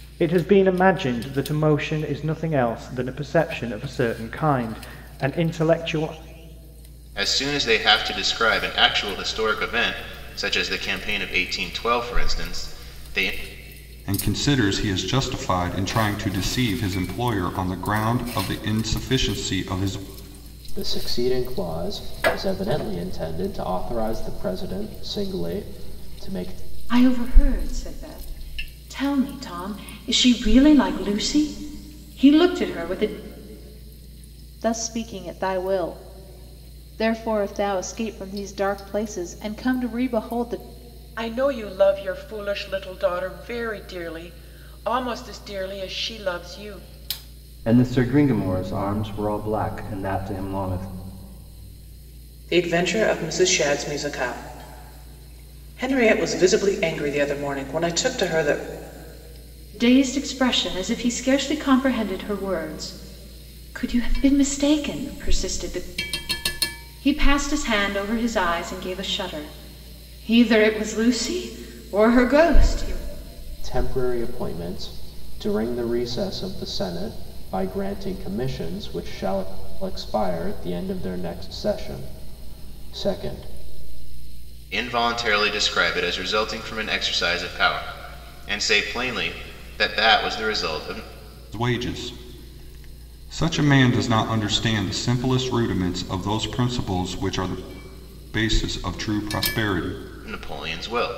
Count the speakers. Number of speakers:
9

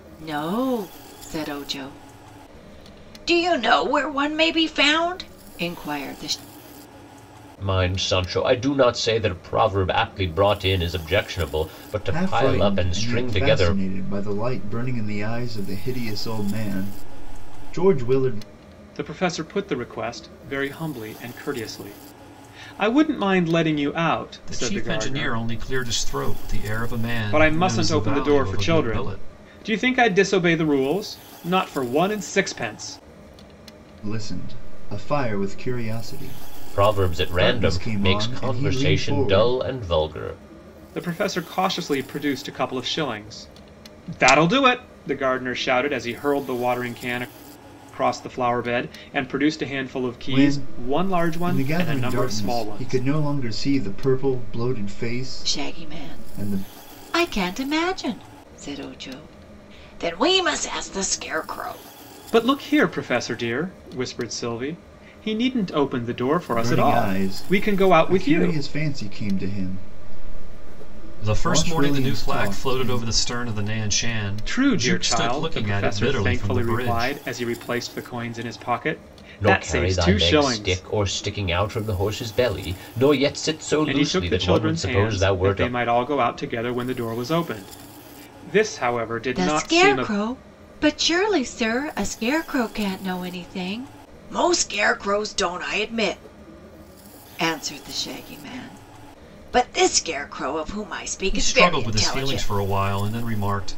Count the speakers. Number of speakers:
5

